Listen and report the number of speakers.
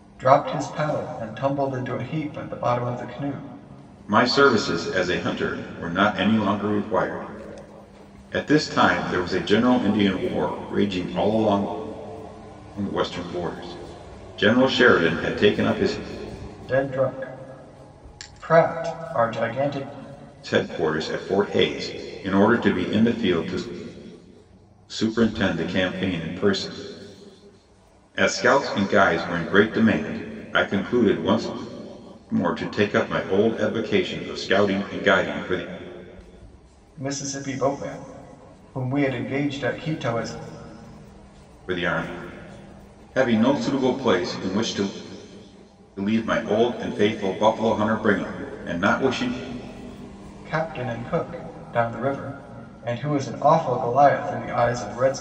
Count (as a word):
two